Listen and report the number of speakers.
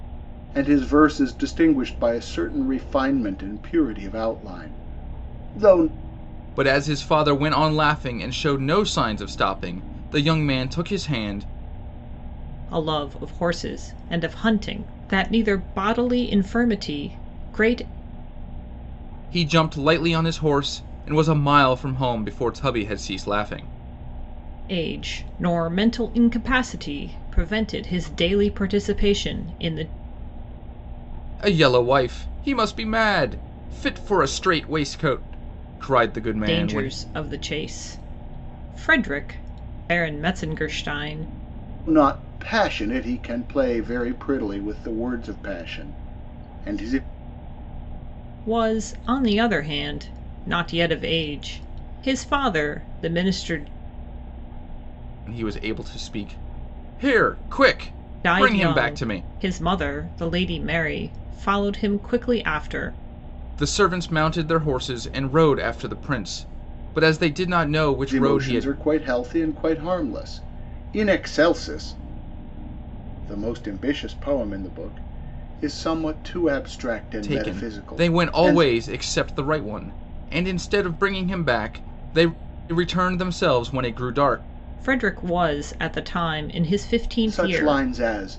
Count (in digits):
3